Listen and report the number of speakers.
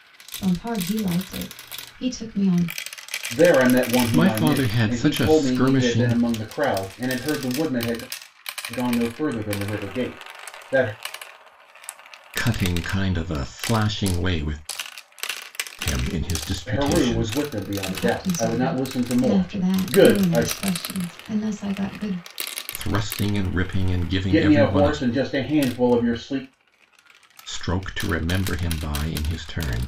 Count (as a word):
three